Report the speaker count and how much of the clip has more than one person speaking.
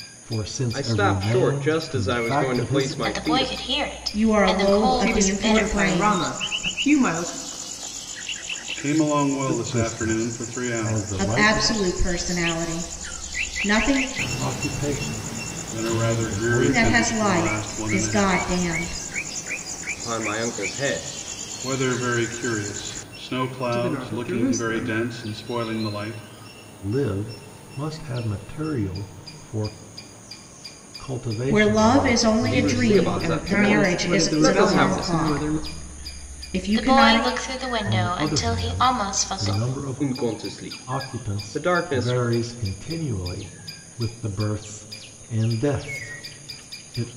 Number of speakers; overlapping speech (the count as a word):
six, about 42%